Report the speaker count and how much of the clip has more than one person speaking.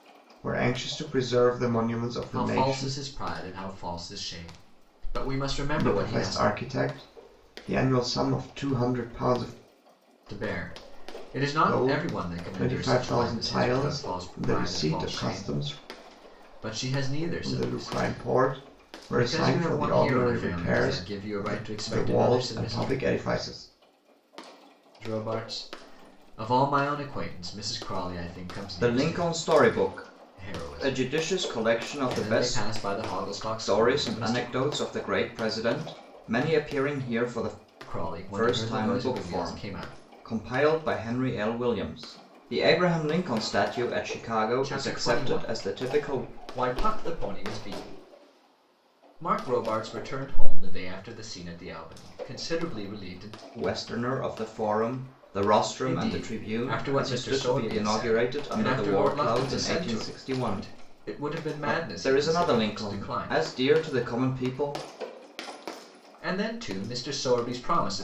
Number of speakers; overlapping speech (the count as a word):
two, about 36%